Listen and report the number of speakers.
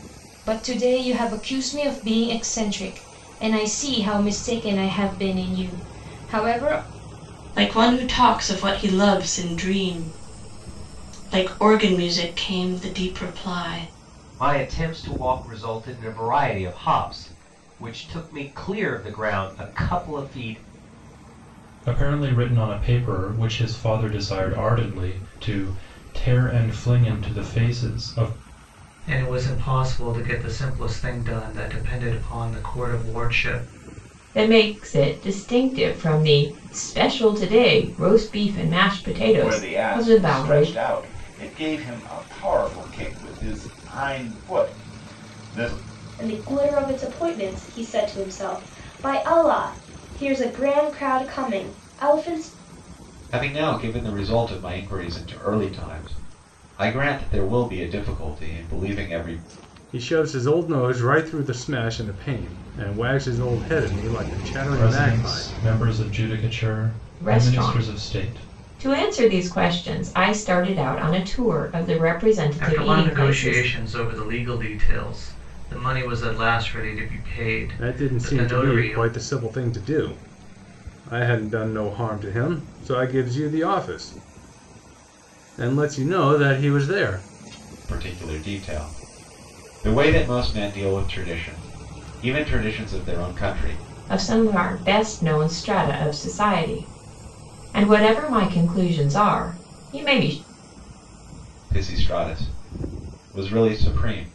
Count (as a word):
ten